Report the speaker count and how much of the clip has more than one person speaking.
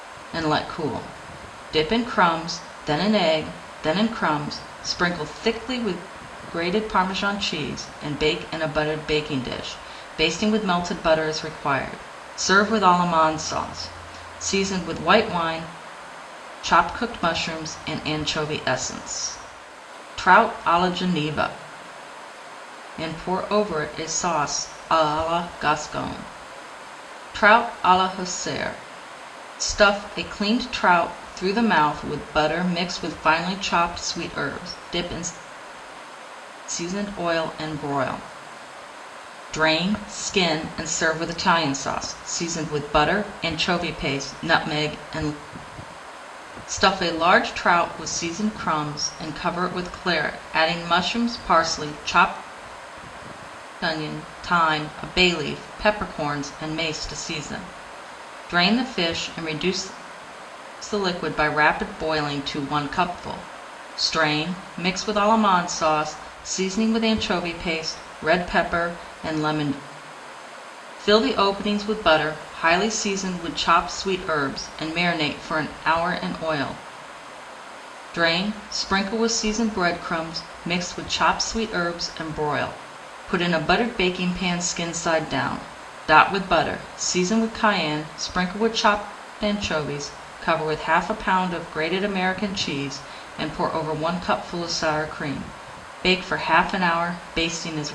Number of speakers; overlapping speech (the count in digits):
1, no overlap